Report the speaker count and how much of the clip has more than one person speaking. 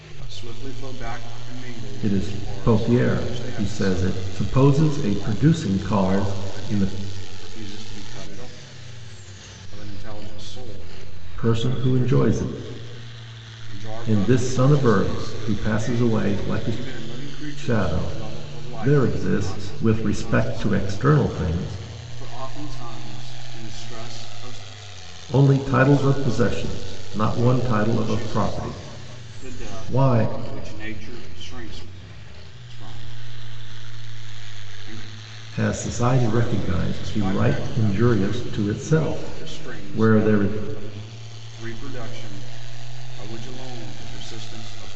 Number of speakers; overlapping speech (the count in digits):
2, about 44%